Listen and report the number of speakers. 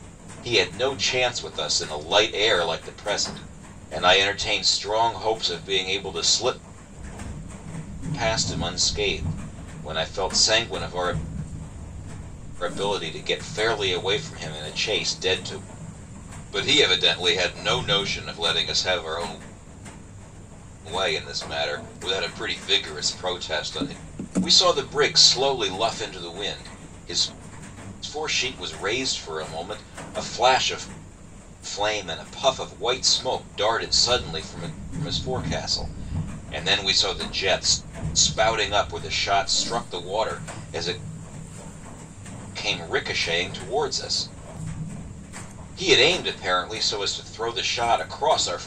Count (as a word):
one